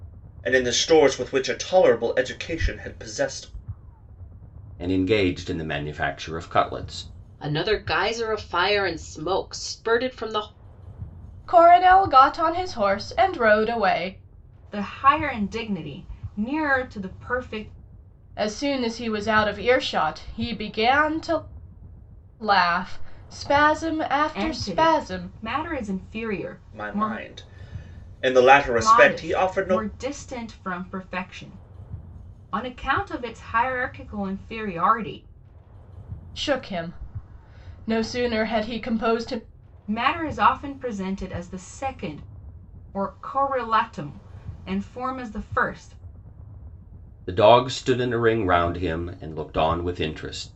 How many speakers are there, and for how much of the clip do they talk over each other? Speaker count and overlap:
5, about 5%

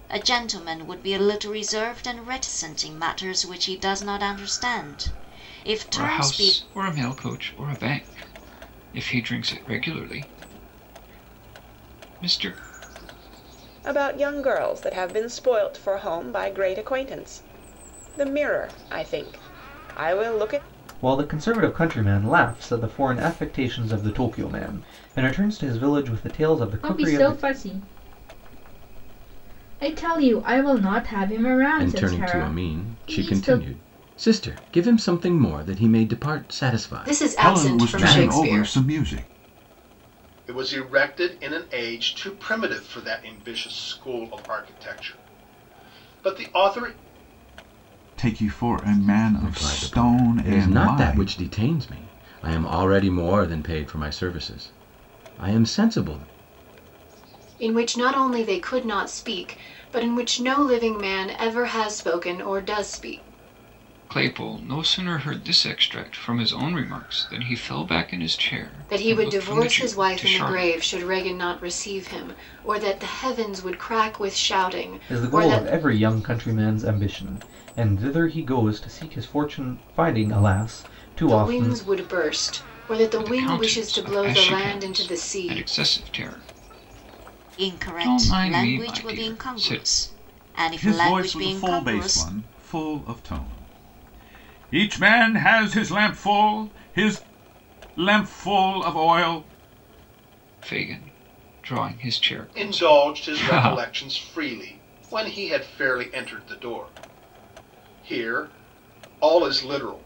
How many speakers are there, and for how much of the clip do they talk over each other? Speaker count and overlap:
9, about 16%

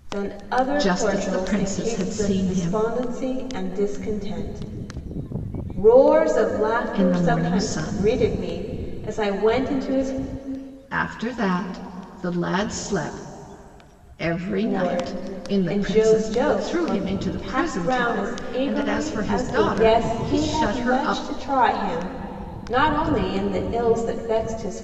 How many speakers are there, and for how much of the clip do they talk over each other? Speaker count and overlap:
2, about 39%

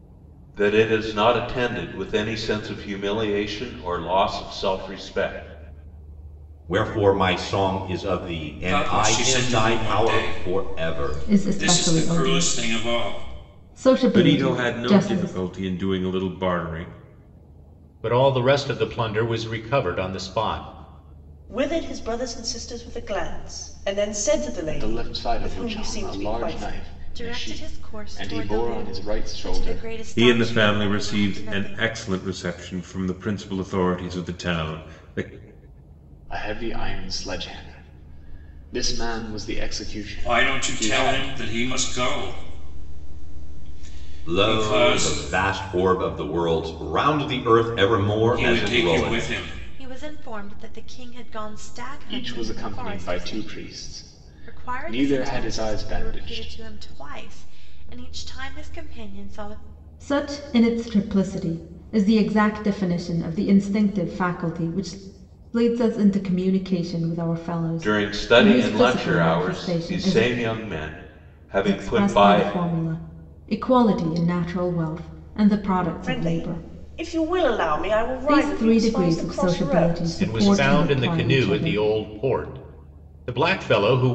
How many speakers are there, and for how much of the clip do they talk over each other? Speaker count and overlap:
9, about 32%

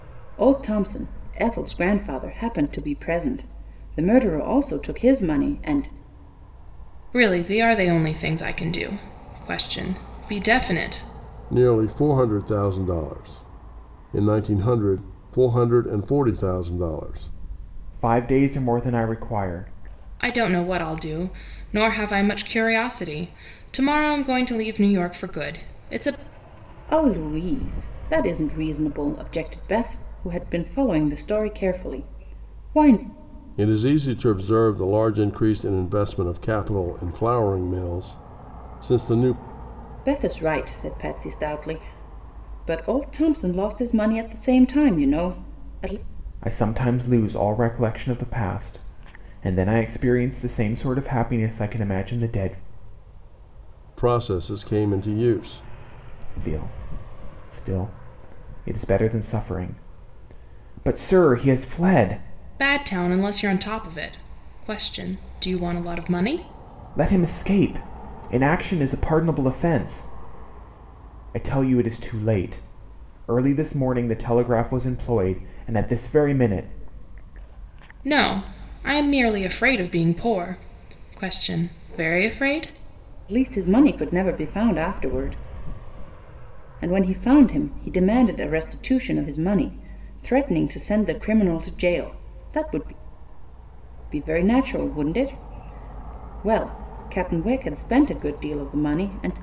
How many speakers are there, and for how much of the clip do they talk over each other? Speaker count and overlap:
4, no overlap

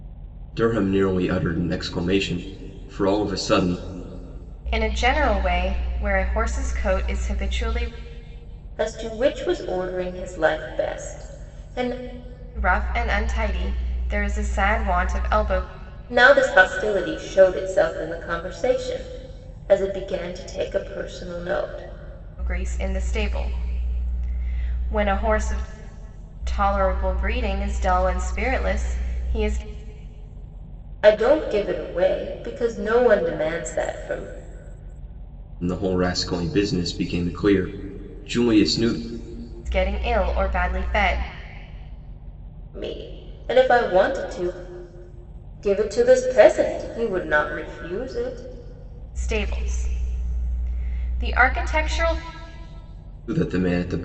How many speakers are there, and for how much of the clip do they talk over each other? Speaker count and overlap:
3, no overlap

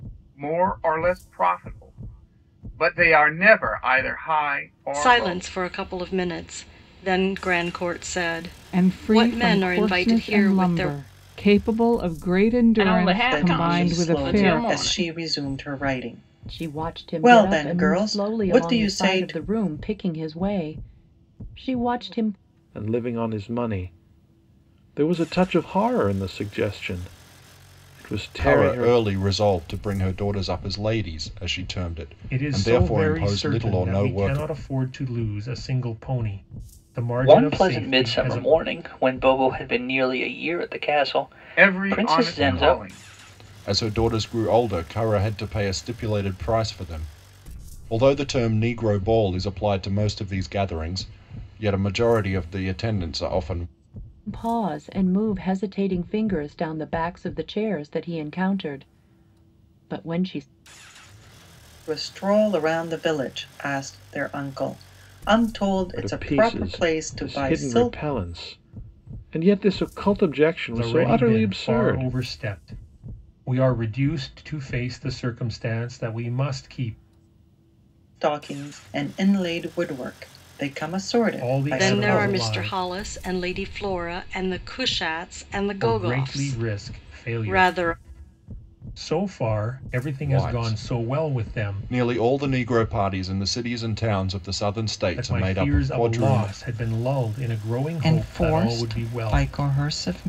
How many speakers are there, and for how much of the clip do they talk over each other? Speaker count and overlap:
10, about 25%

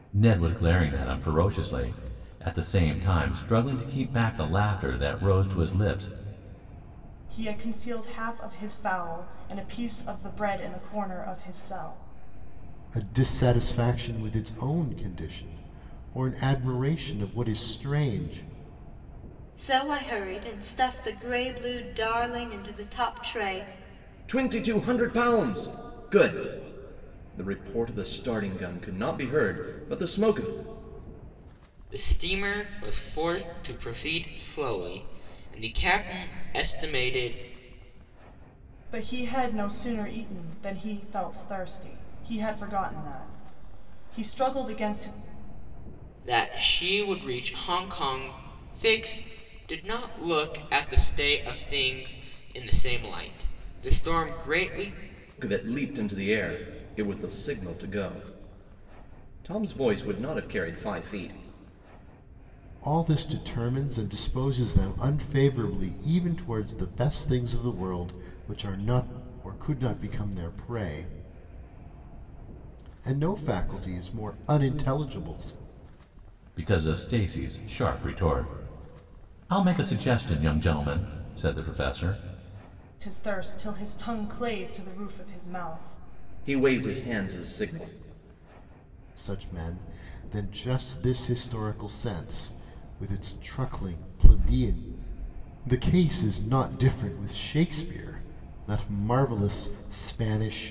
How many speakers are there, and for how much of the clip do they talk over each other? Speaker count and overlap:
6, no overlap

